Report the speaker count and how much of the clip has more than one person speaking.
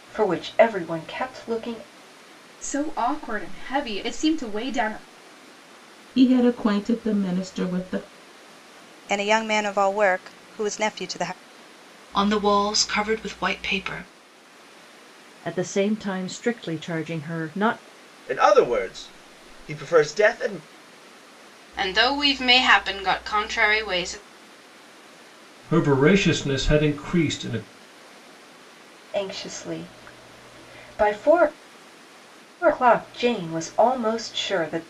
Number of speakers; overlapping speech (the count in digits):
9, no overlap